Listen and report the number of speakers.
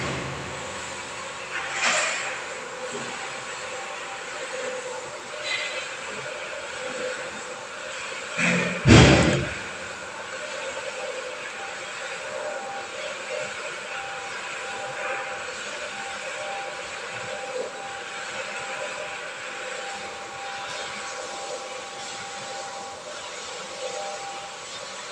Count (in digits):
0